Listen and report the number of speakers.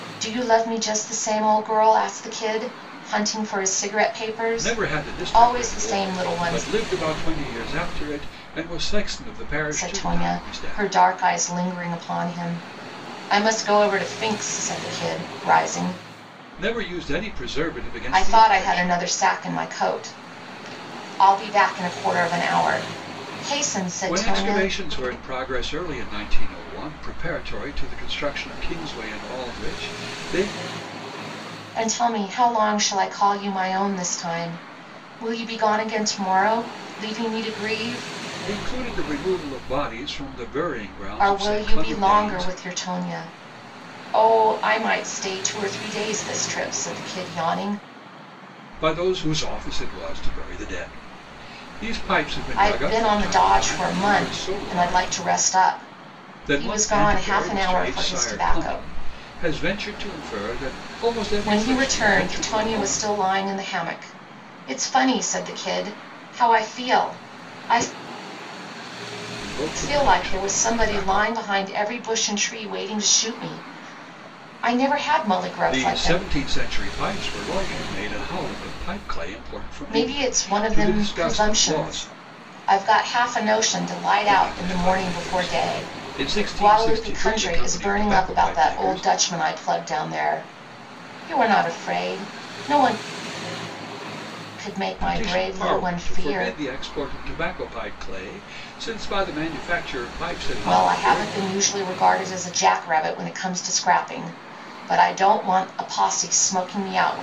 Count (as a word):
two